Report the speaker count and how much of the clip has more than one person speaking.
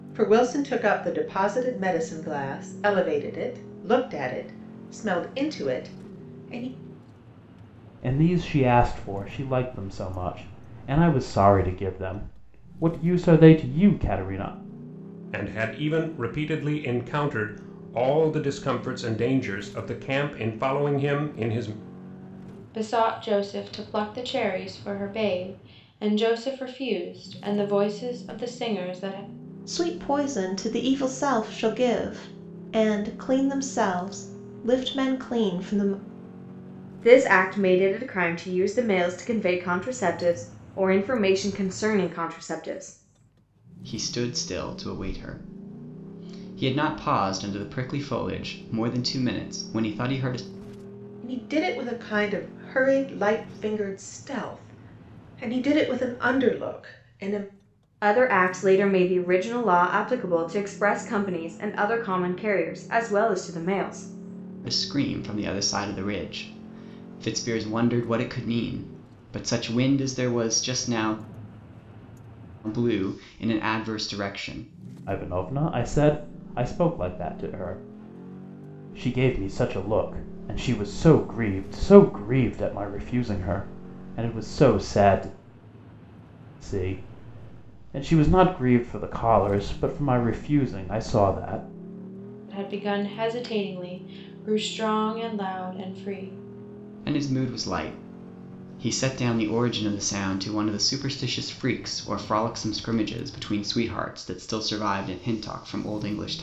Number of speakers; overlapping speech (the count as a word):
seven, no overlap